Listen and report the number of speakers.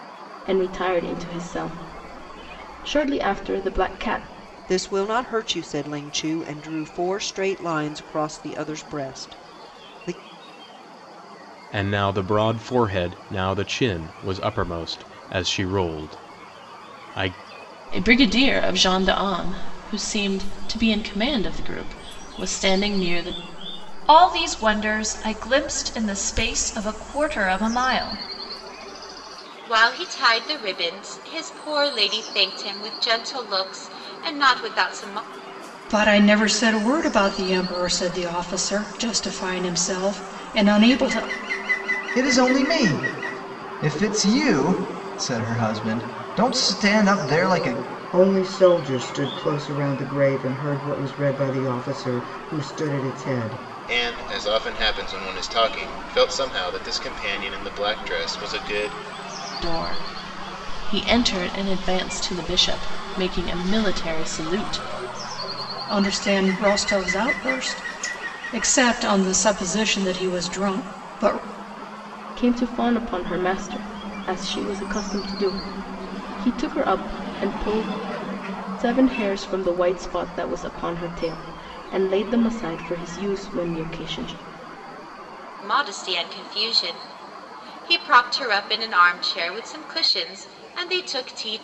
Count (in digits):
10